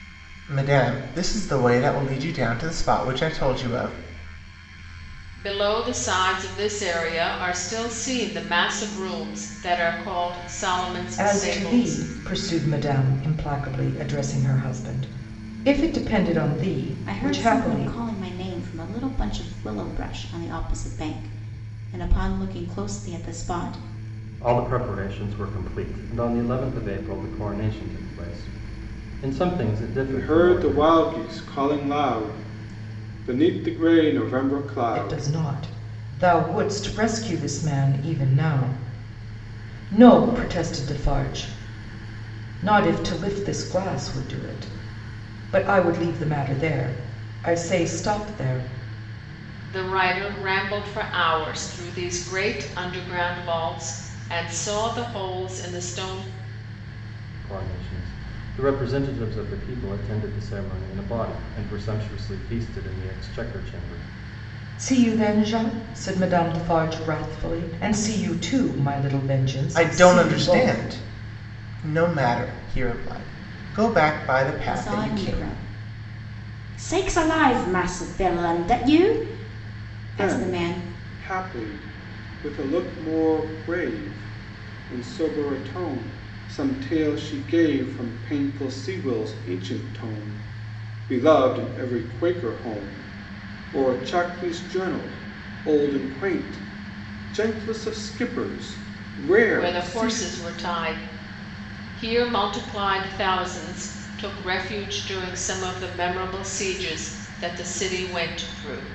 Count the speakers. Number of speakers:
6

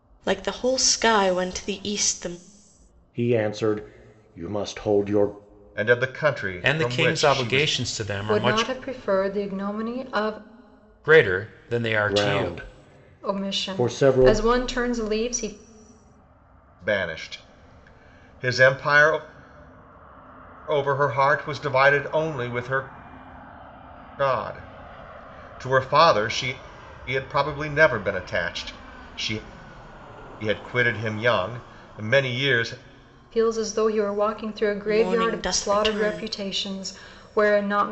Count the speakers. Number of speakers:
5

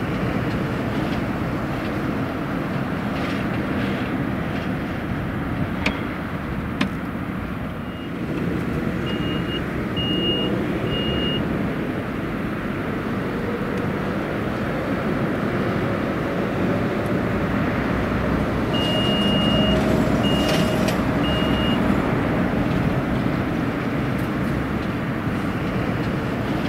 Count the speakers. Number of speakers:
0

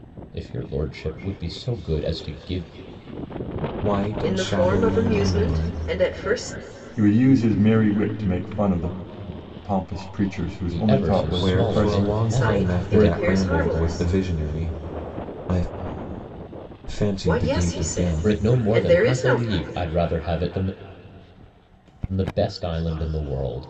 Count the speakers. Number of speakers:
4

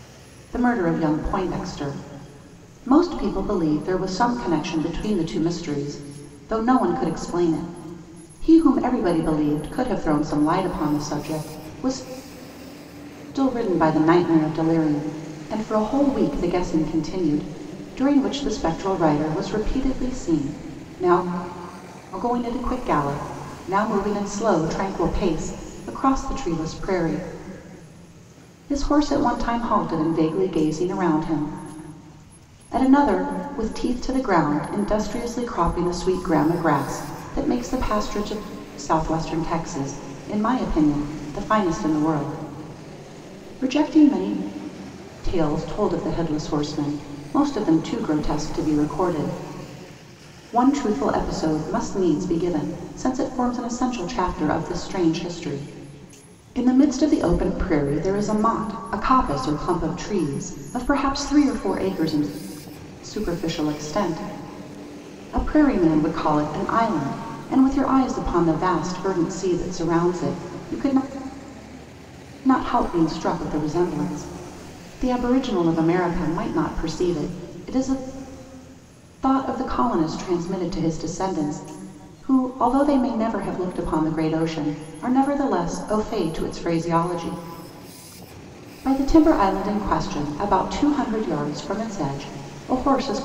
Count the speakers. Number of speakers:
1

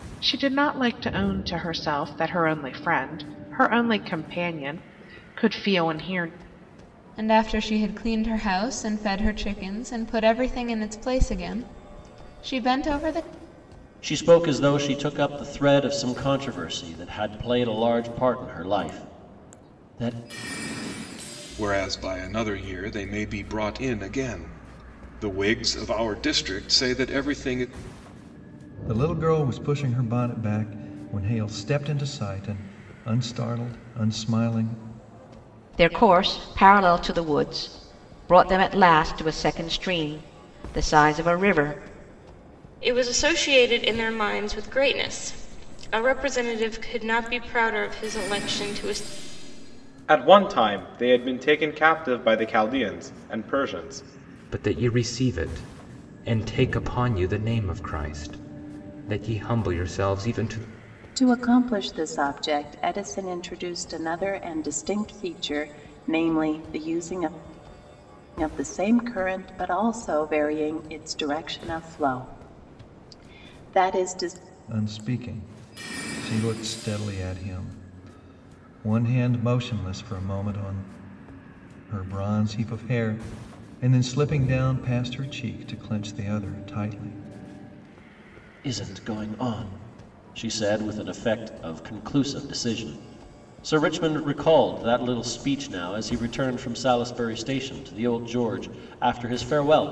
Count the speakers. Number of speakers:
10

